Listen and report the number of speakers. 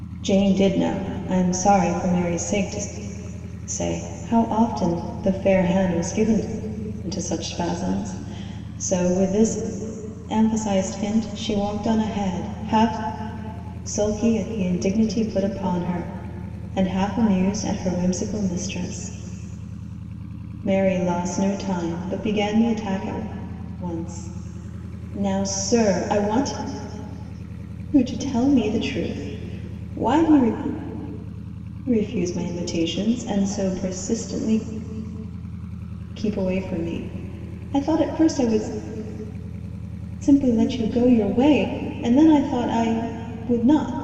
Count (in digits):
1